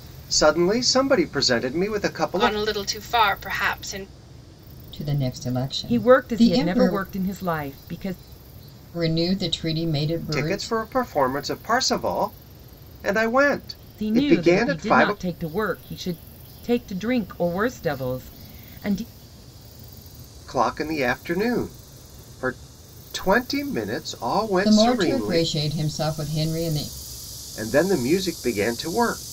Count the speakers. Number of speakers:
4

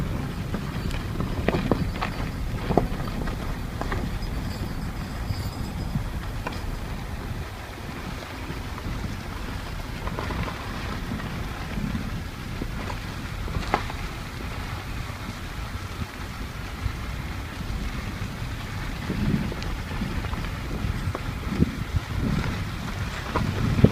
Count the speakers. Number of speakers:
0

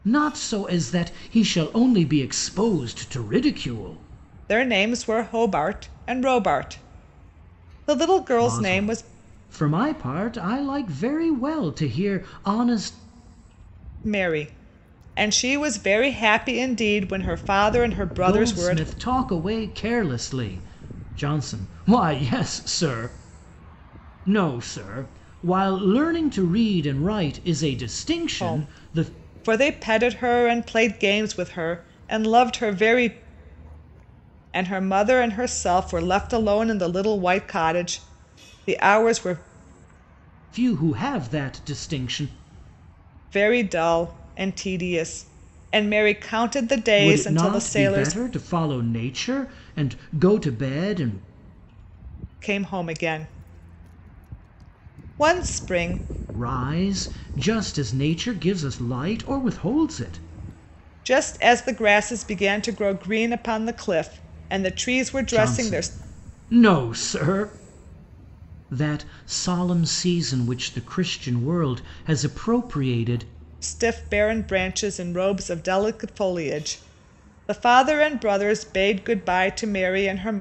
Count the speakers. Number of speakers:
2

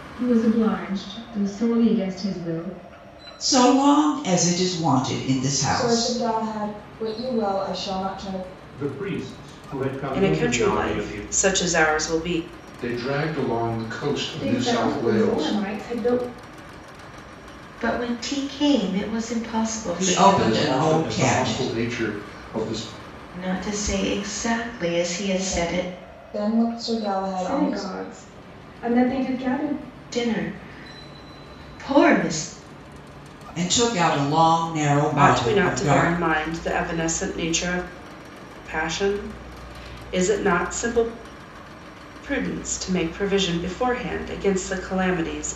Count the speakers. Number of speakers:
8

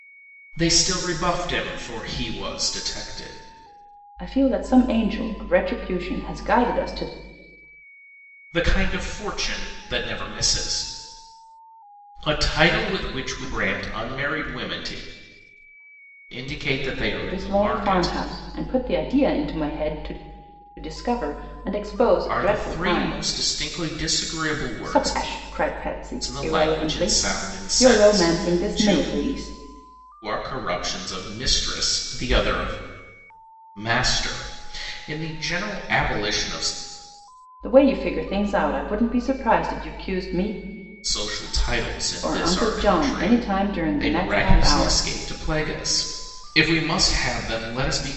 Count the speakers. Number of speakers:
2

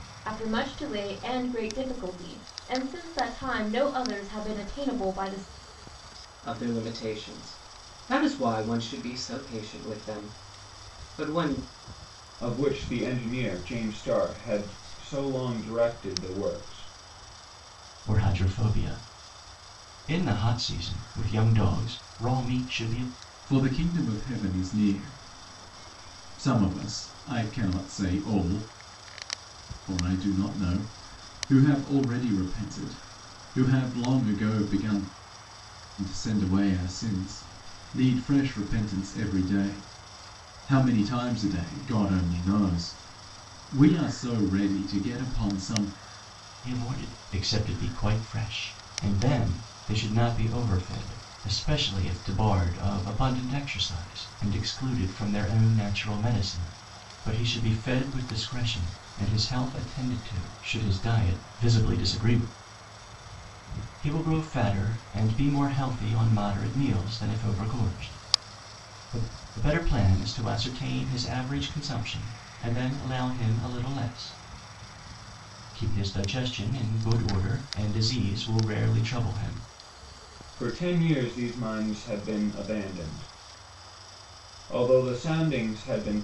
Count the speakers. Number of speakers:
5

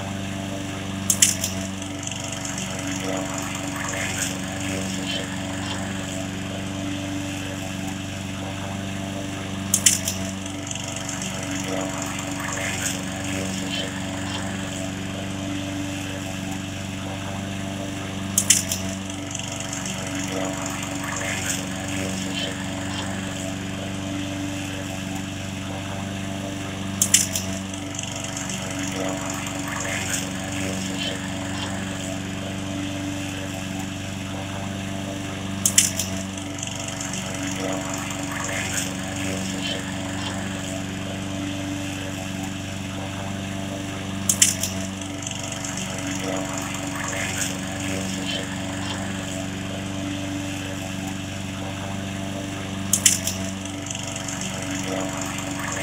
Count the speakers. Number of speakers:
0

